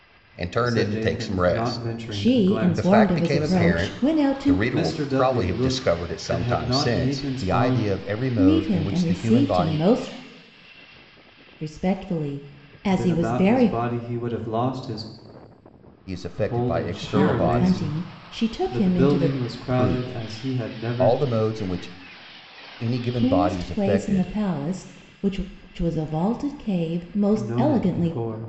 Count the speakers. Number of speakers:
3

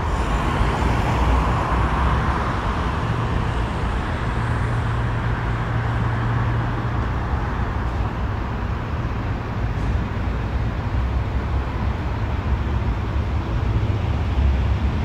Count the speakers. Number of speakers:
0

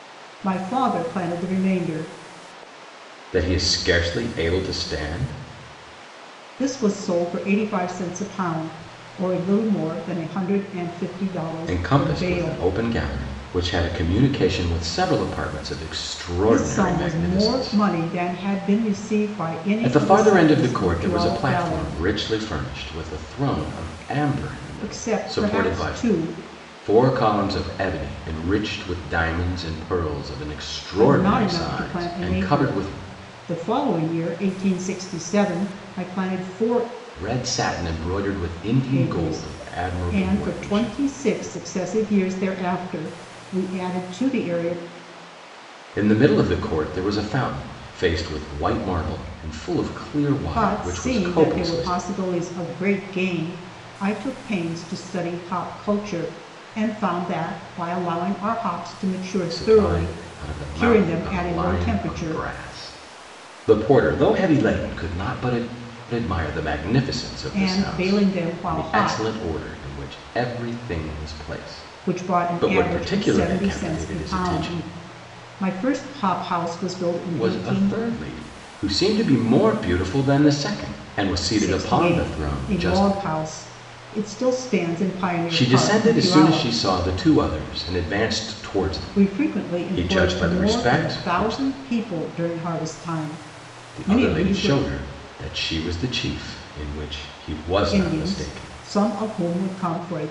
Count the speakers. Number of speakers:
2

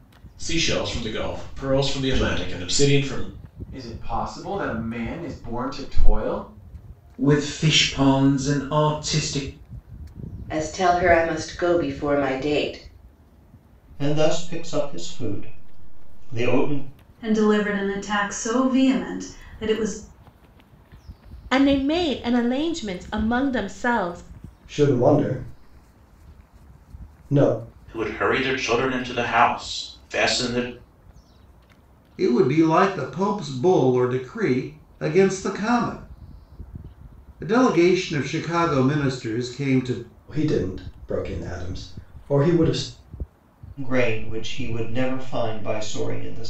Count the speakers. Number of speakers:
10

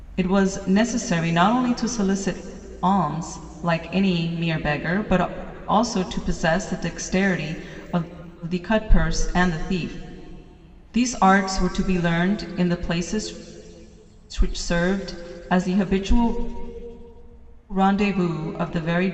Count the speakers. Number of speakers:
1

